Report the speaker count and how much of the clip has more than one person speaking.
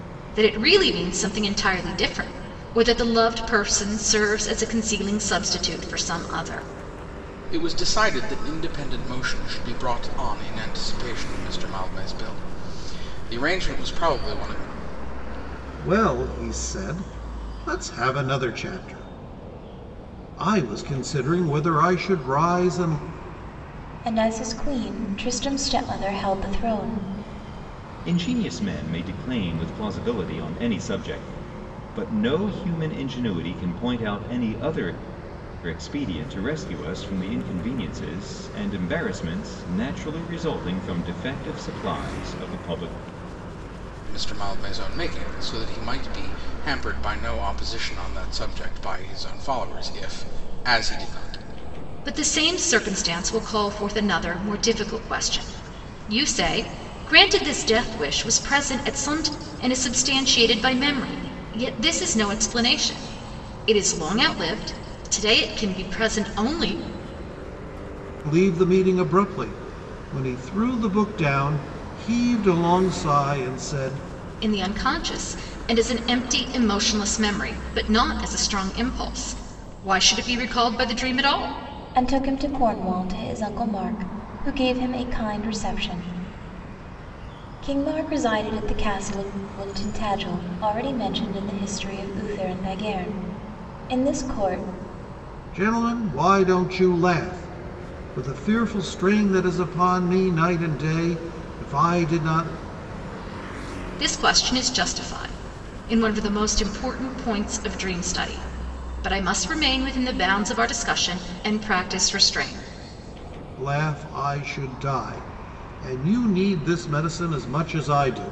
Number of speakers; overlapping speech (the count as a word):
five, no overlap